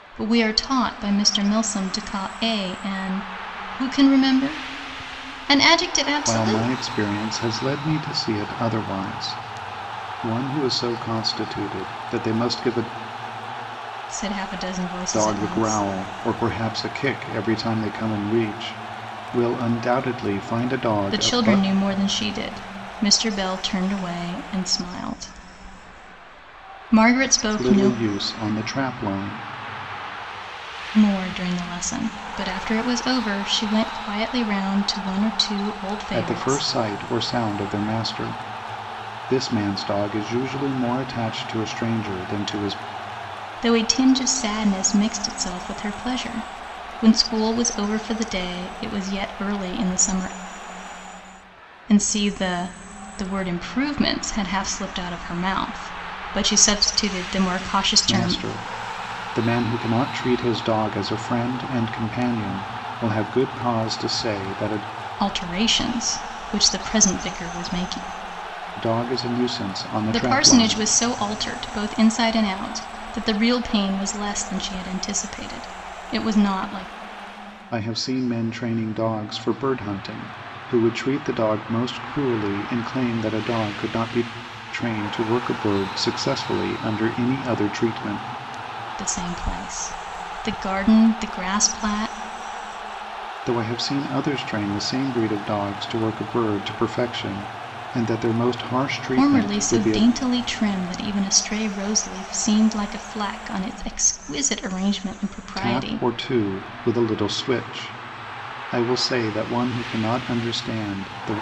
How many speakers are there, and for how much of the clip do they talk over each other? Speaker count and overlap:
2, about 5%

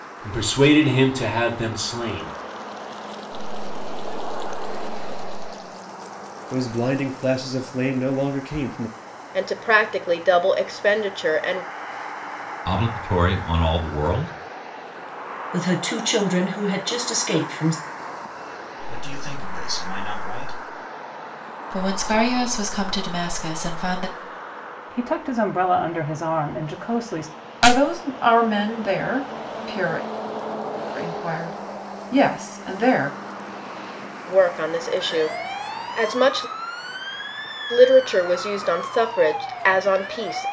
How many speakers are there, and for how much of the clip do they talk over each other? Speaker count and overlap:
10, no overlap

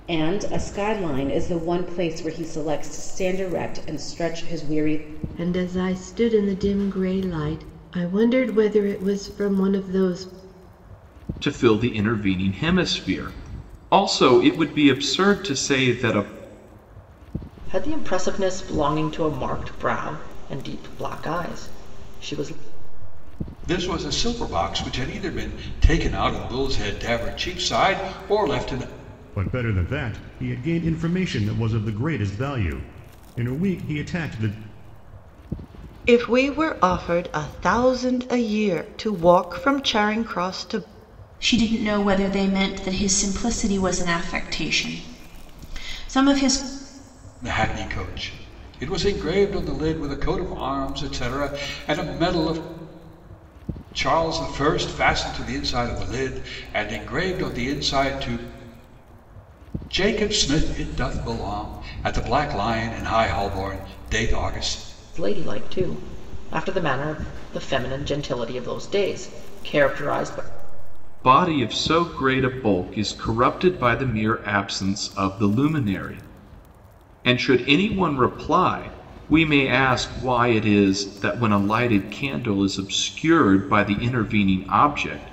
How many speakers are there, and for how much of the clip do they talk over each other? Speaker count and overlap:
8, no overlap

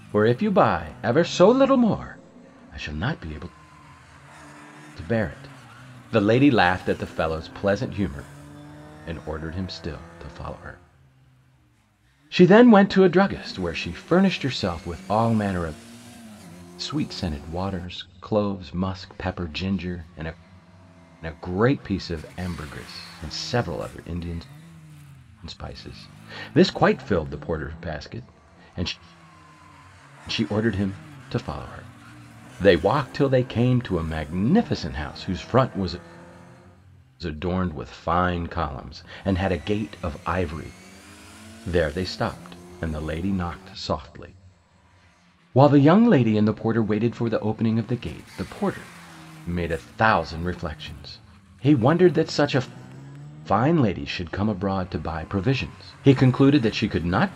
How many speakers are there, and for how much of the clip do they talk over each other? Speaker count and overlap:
1, no overlap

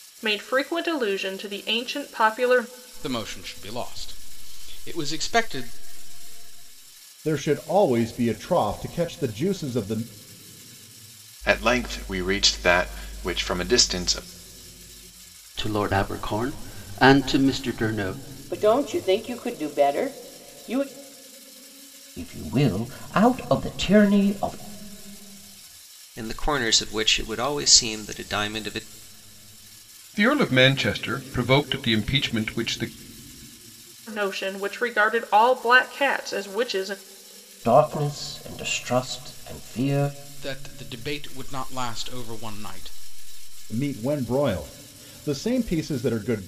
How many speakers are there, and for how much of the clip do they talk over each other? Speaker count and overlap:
9, no overlap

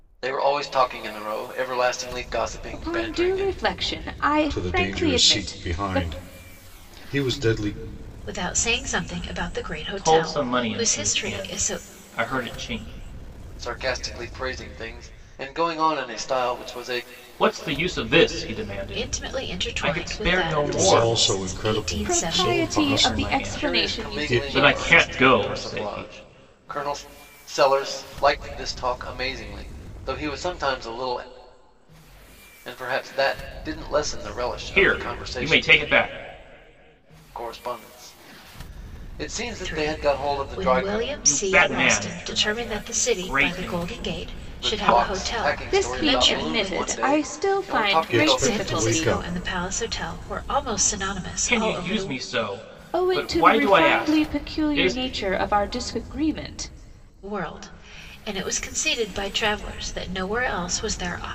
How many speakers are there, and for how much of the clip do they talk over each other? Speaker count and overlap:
5, about 41%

